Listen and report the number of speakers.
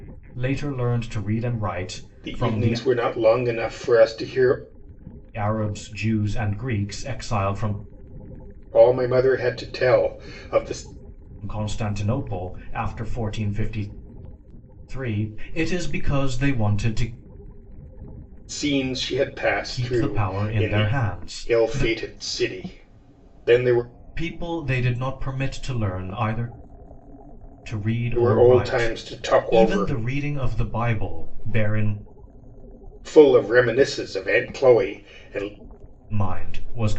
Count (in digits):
2